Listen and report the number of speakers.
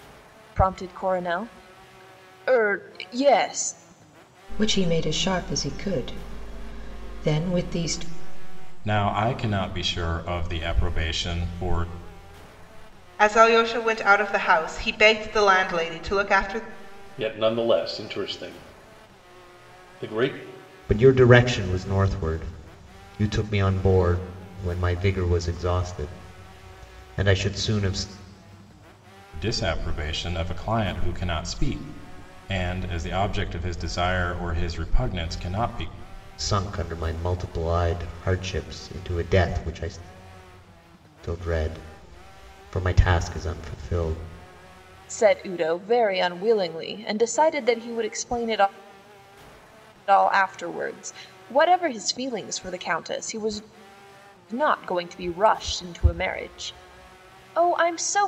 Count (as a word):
six